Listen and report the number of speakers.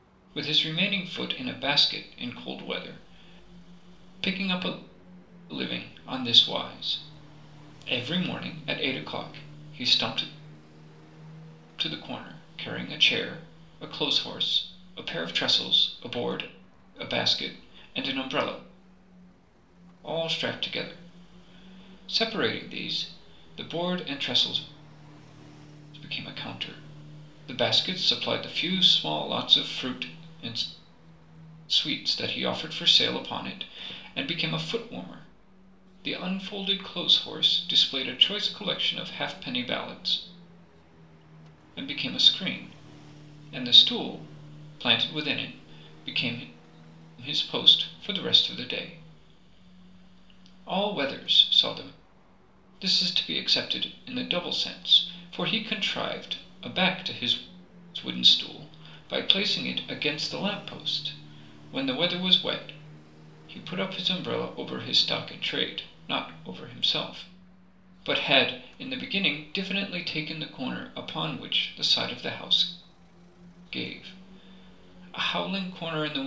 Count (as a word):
one